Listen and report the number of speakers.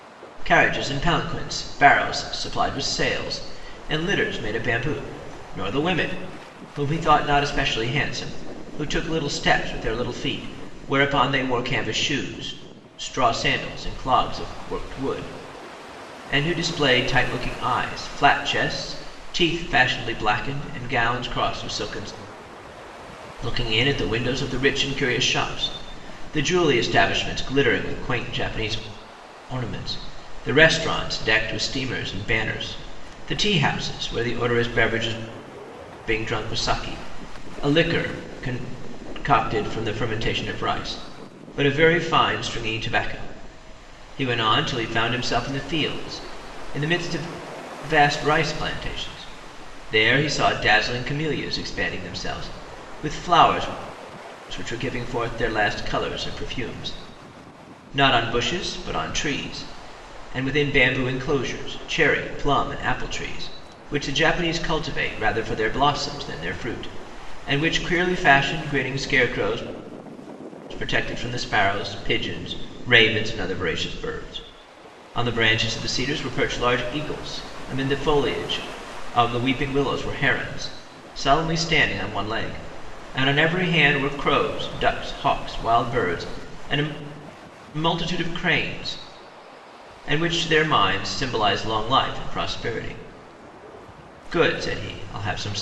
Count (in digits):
1